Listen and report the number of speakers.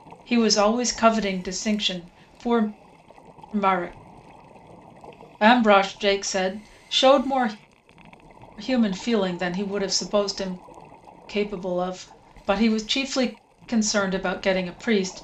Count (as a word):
one